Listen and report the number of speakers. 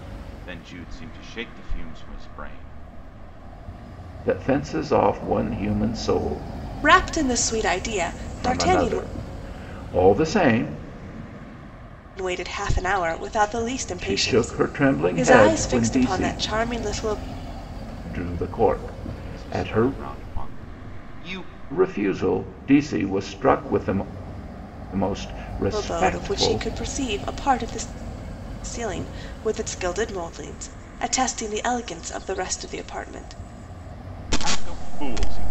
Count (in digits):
3